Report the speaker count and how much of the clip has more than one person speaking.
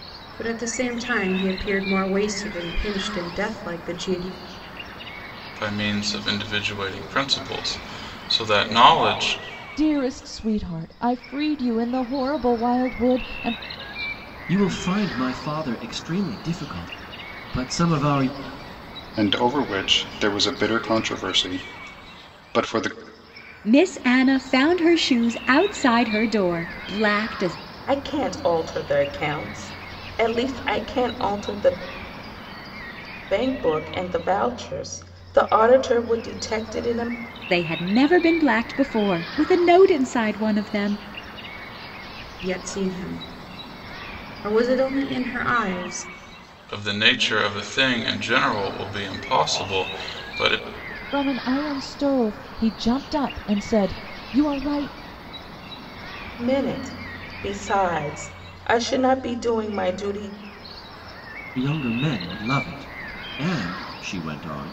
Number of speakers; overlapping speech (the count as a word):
seven, no overlap